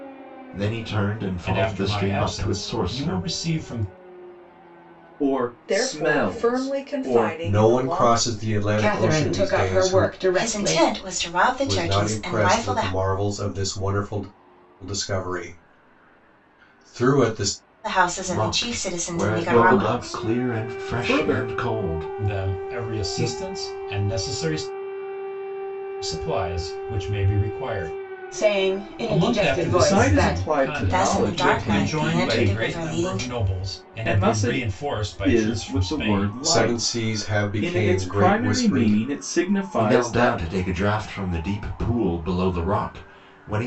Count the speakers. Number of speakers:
7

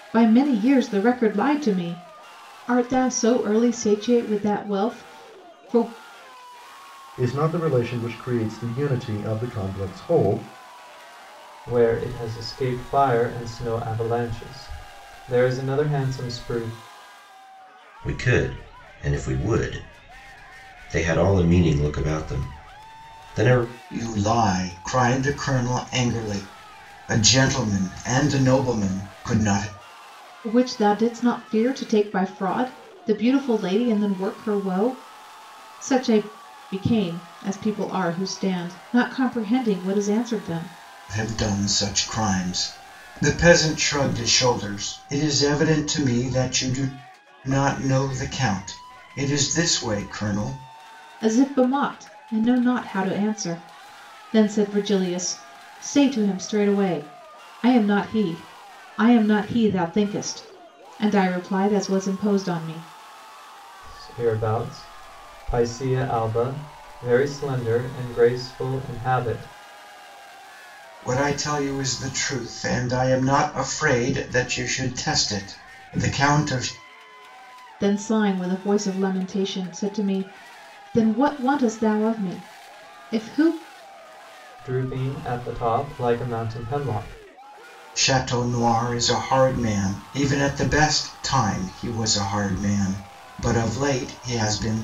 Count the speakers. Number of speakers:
5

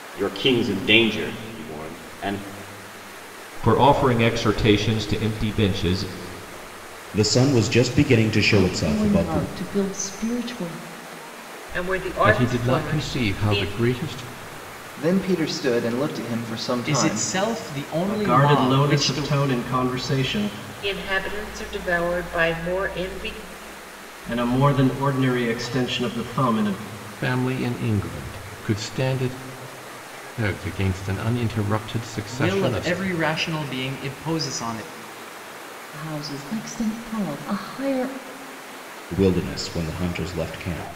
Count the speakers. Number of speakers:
9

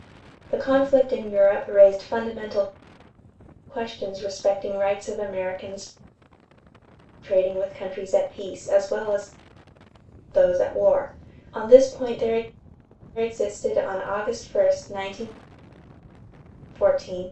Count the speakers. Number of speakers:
1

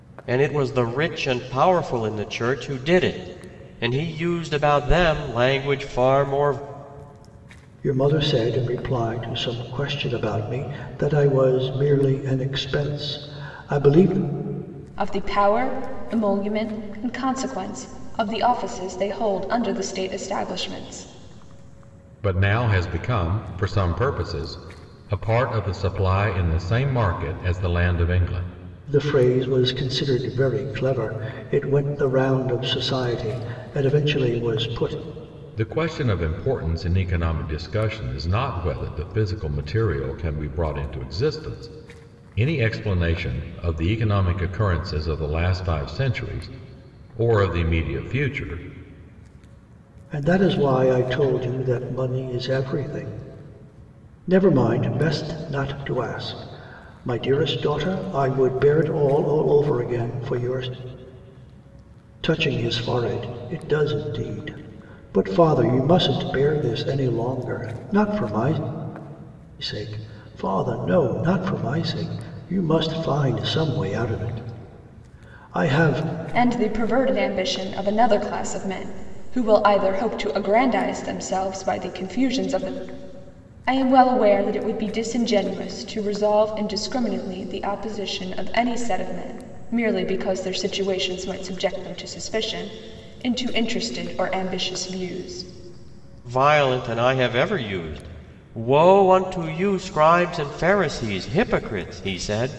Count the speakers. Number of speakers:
4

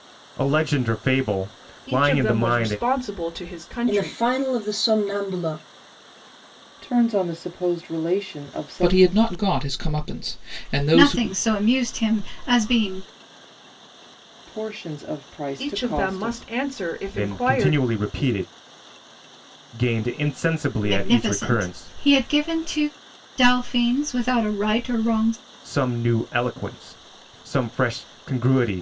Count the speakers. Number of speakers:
6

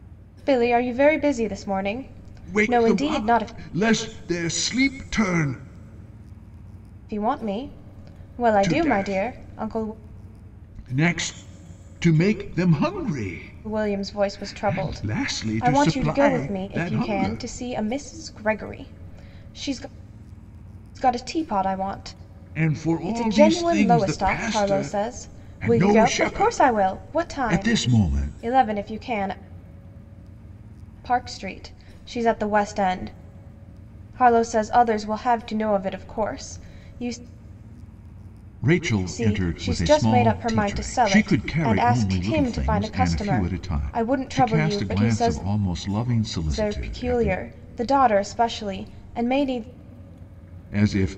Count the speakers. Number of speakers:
2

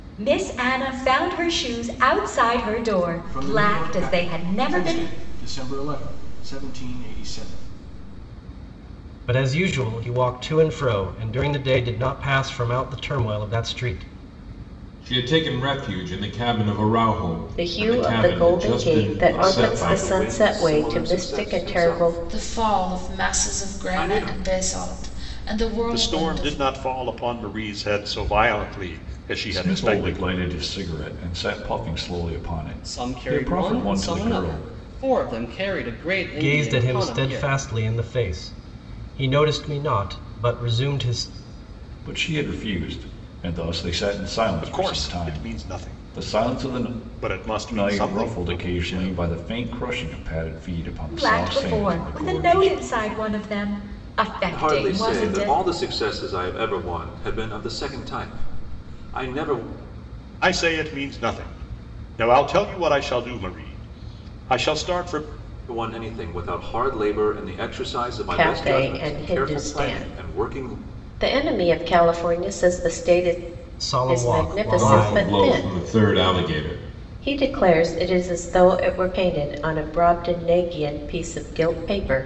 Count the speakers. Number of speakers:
10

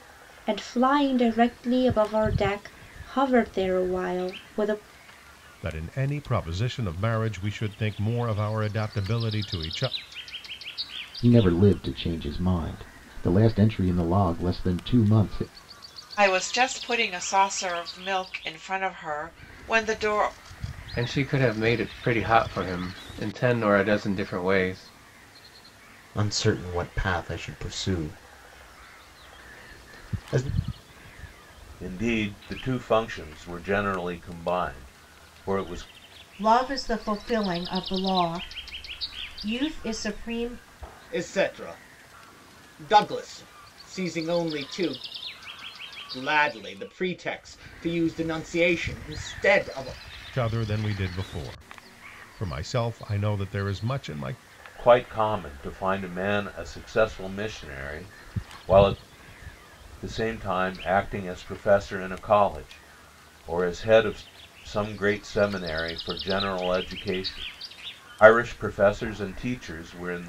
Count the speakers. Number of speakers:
9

